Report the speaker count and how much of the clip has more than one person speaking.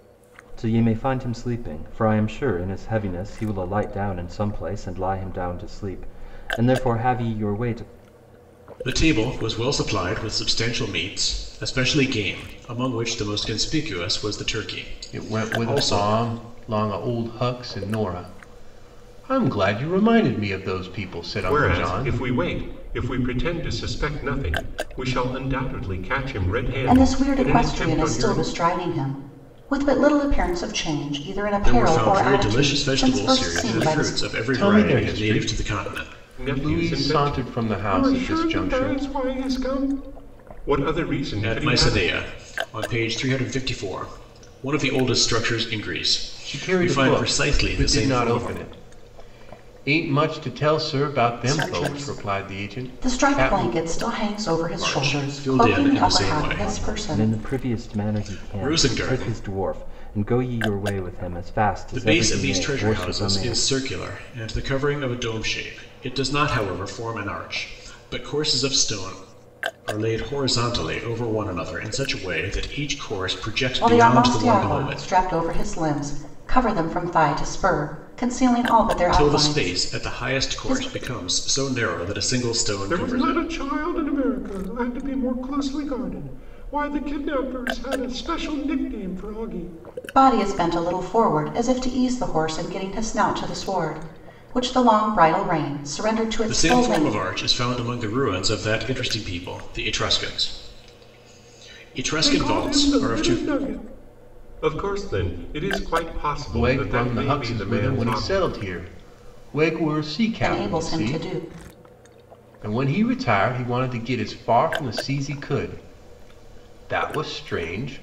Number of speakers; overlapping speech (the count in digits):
5, about 26%